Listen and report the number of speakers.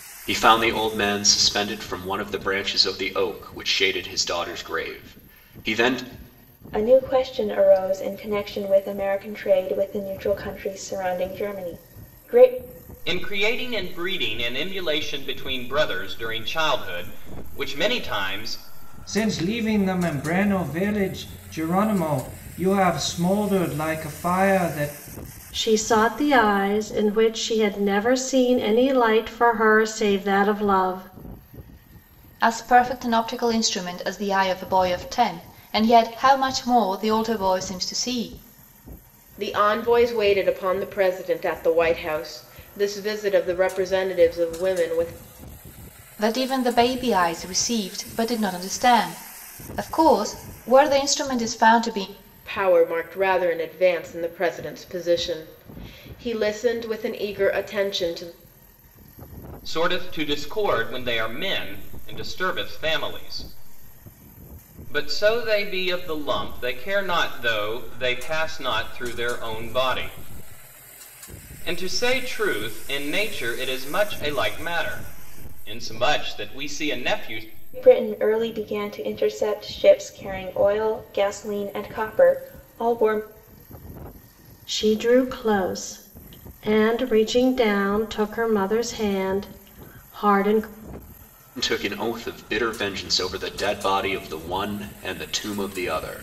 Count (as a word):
seven